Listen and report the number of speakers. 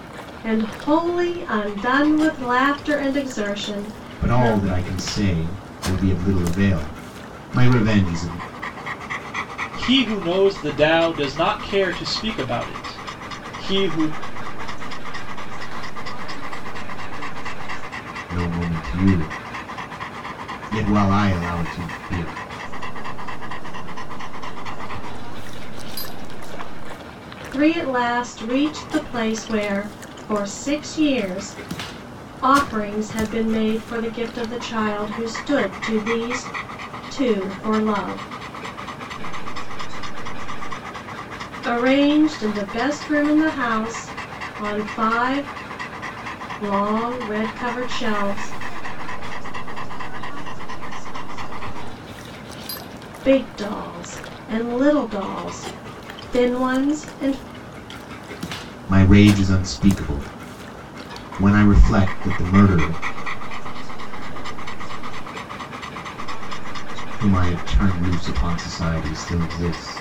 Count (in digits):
4